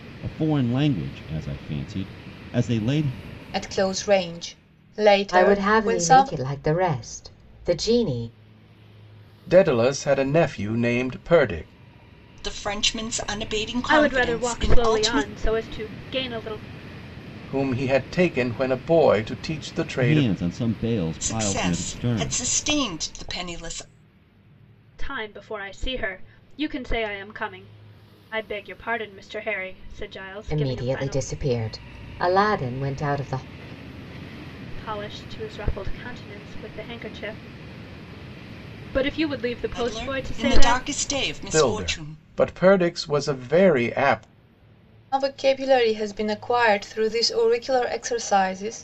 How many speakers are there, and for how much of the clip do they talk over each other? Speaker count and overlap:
six, about 14%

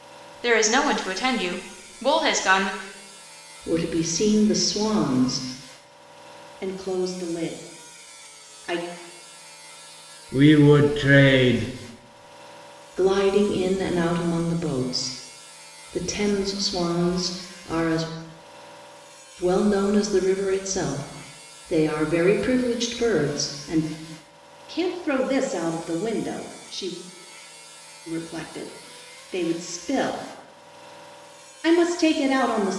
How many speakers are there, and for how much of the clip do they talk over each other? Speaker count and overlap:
four, no overlap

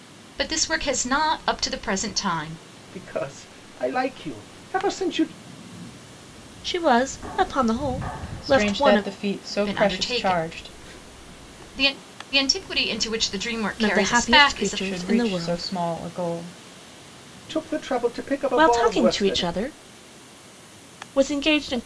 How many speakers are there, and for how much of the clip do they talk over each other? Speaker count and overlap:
four, about 22%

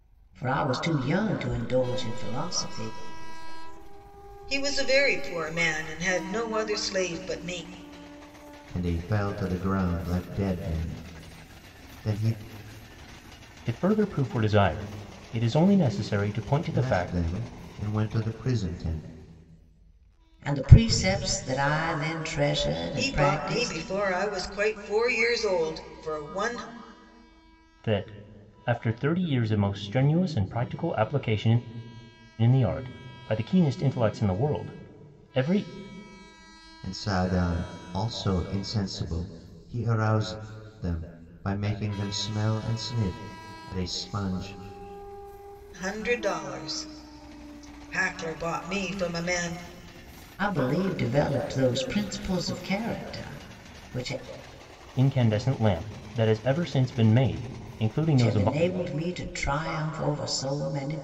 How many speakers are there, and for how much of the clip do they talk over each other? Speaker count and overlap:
five, about 7%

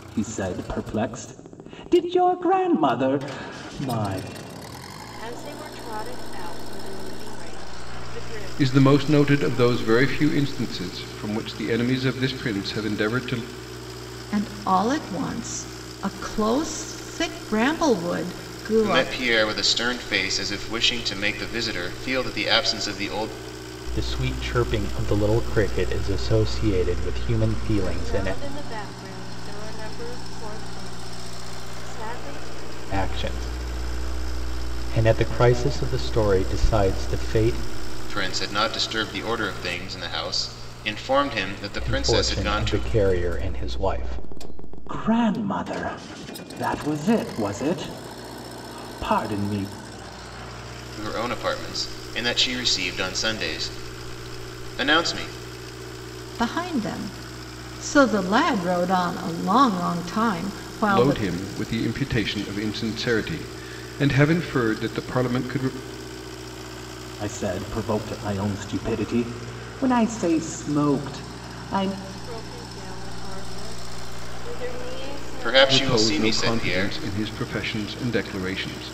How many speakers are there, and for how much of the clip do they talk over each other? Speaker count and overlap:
six, about 7%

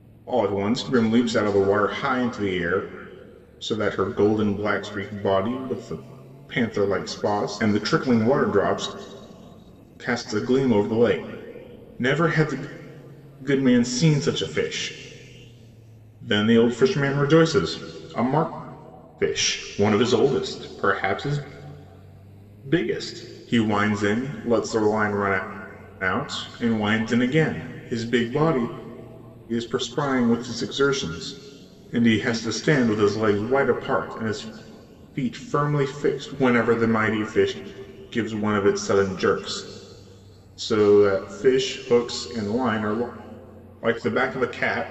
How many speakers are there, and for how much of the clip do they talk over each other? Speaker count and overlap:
one, no overlap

